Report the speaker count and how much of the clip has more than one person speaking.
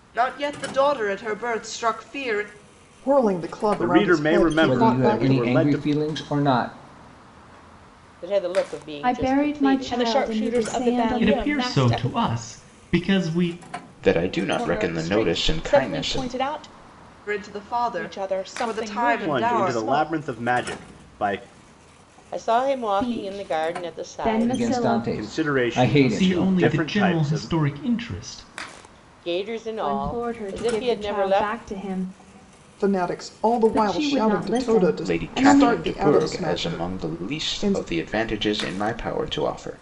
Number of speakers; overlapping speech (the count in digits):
9, about 50%